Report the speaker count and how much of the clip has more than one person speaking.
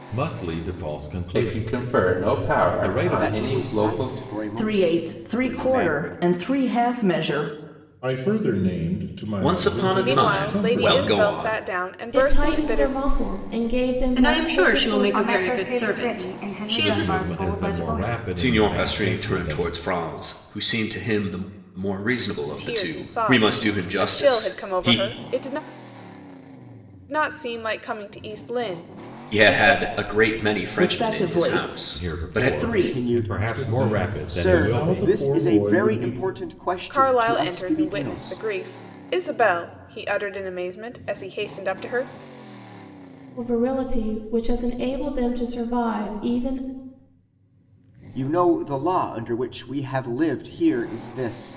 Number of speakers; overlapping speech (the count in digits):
10, about 44%